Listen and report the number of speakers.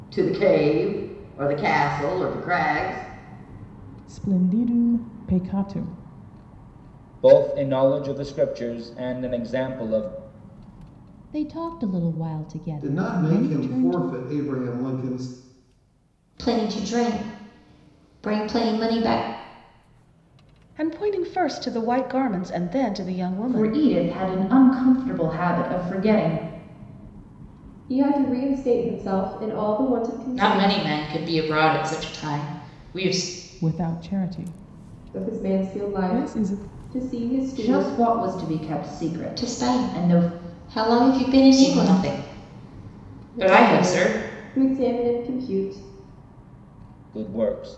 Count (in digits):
10